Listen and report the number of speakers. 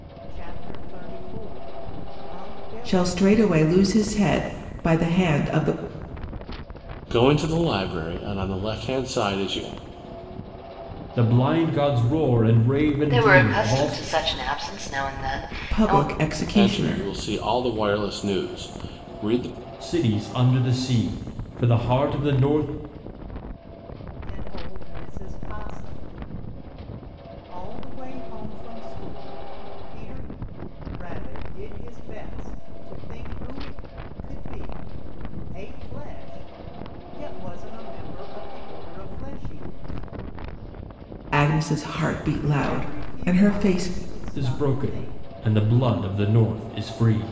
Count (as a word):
five